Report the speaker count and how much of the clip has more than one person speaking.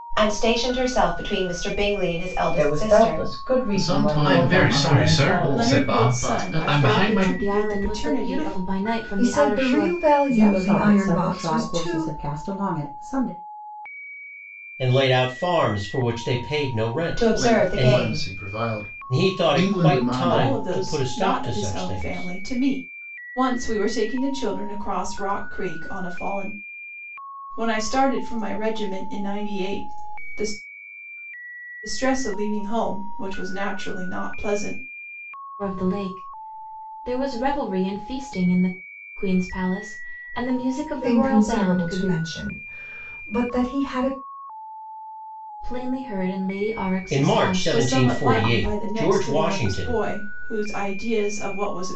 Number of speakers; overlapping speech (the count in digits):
9, about 32%